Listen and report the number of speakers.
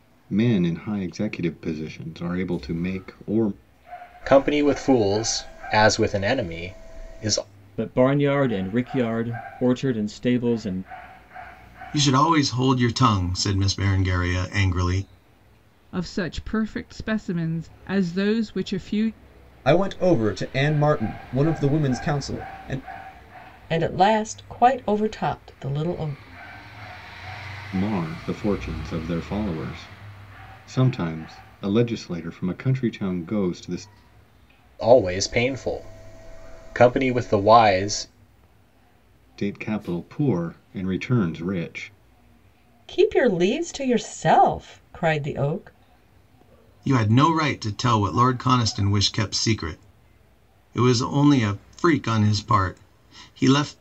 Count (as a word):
seven